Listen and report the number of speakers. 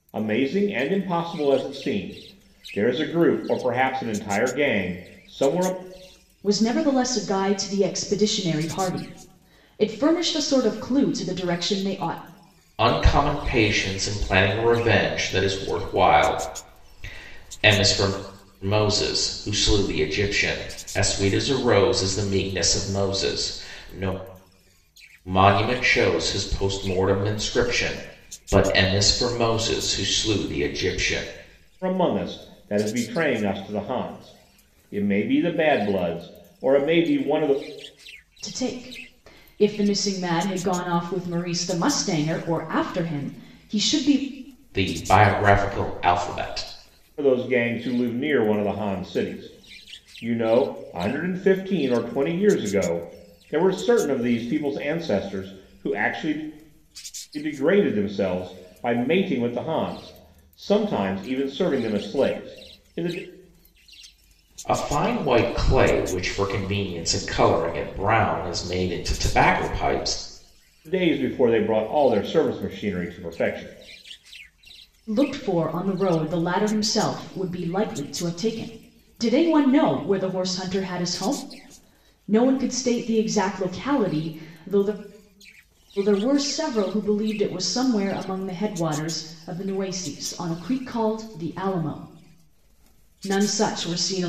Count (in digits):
3